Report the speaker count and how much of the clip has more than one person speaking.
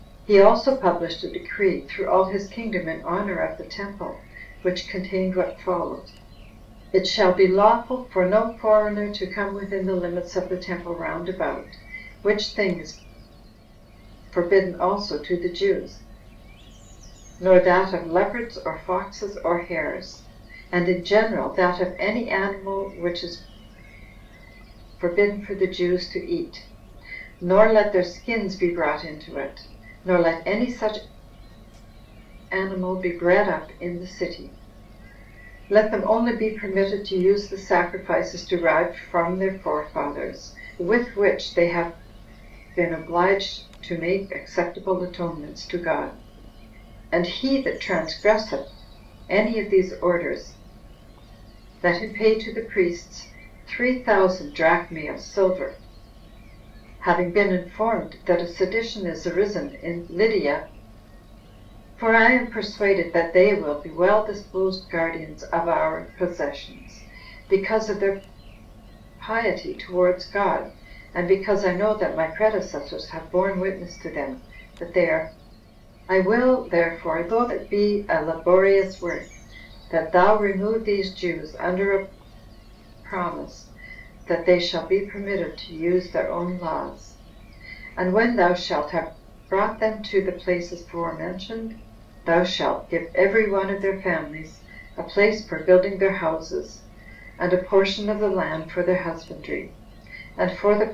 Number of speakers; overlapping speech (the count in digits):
1, no overlap